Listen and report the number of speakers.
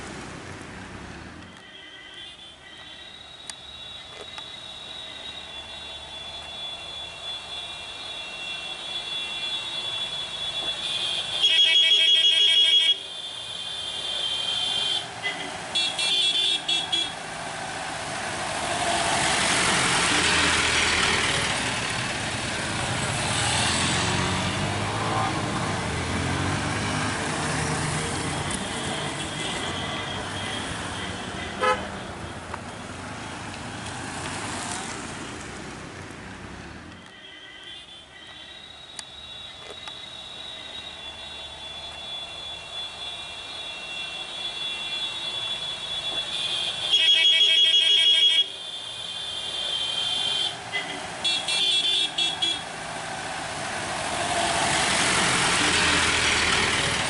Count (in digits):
0